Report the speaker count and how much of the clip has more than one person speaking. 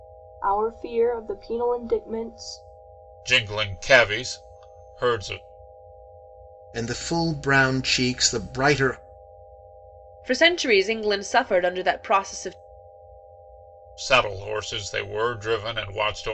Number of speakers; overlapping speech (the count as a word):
four, no overlap